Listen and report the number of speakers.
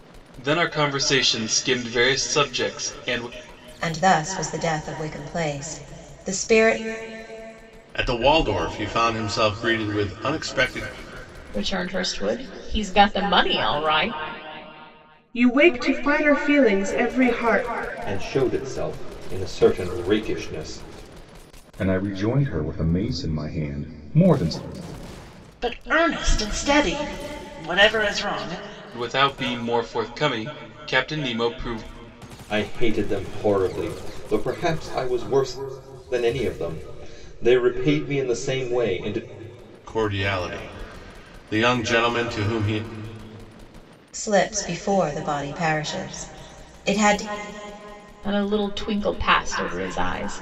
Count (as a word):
eight